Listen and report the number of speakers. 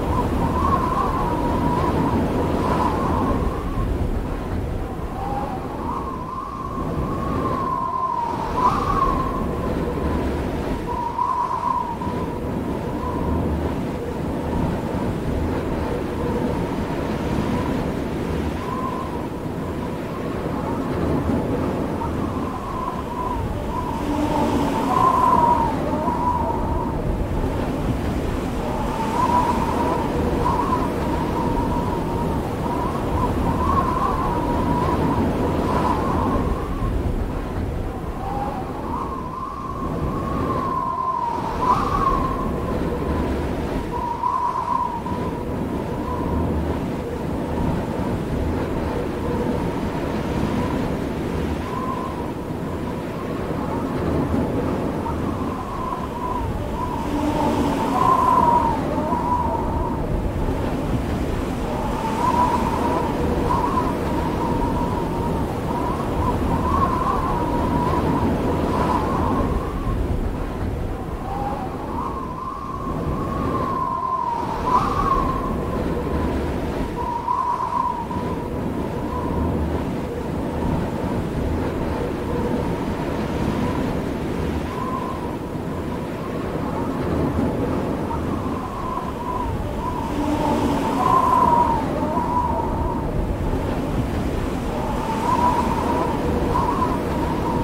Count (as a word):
zero